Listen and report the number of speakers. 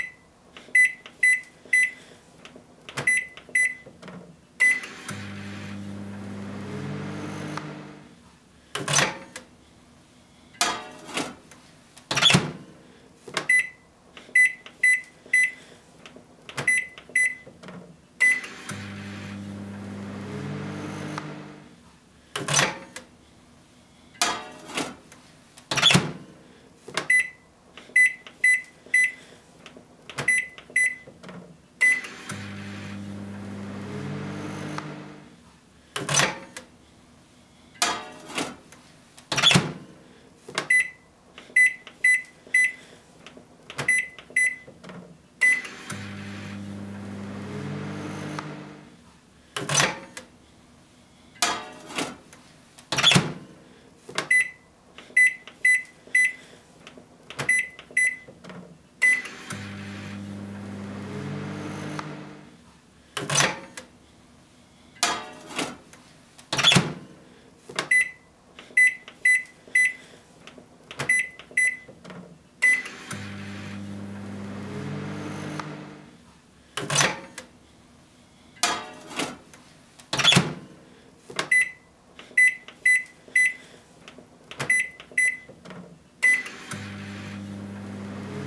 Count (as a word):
zero